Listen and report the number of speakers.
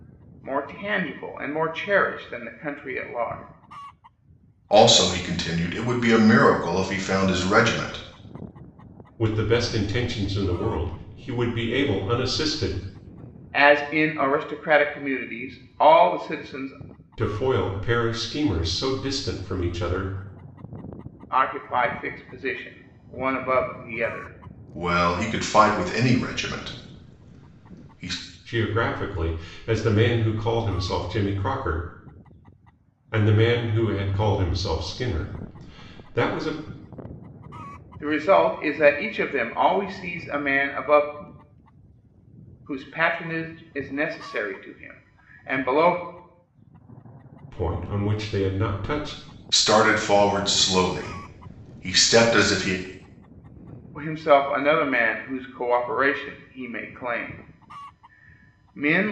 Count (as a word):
three